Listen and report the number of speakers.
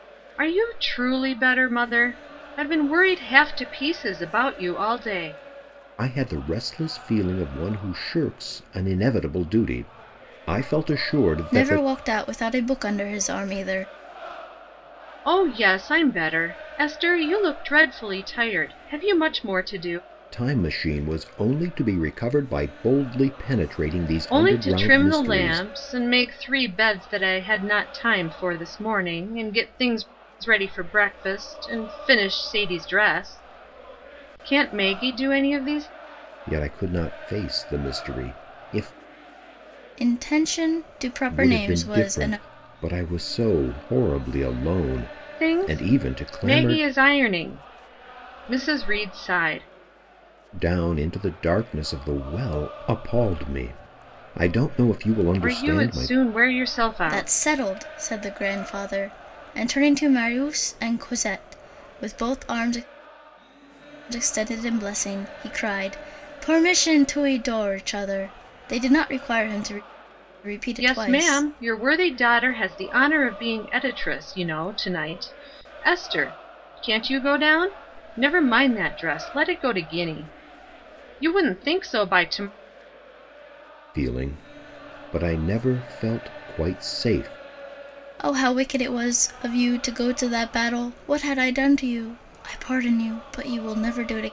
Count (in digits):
3